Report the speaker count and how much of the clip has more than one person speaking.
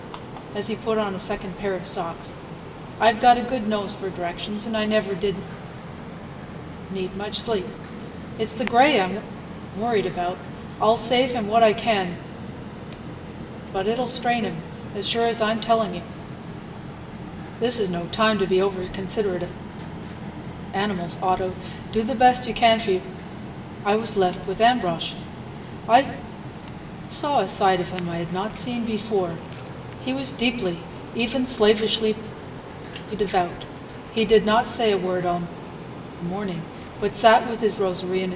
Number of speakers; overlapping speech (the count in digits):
1, no overlap